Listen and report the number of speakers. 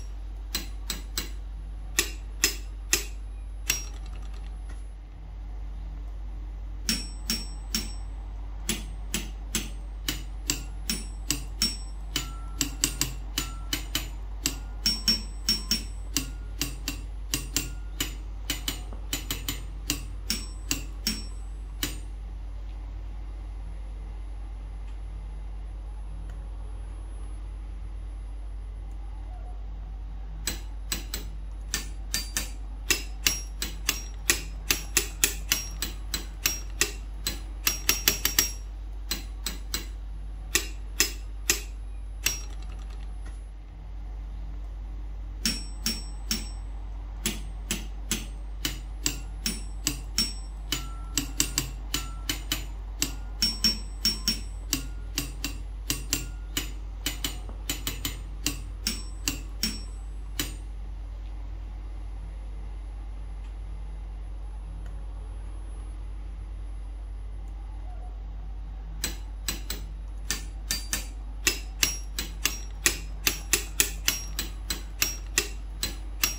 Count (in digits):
0